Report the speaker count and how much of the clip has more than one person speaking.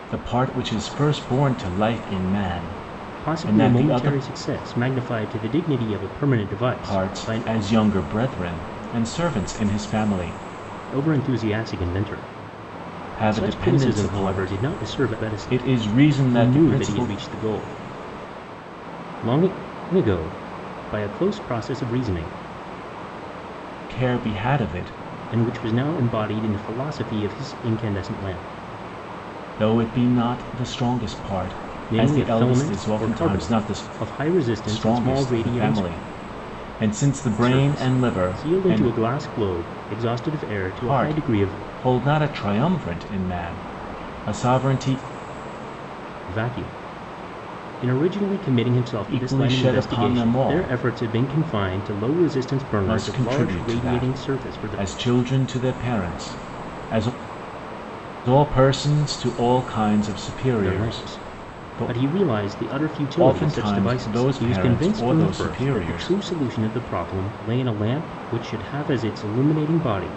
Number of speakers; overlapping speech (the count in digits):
2, about 28%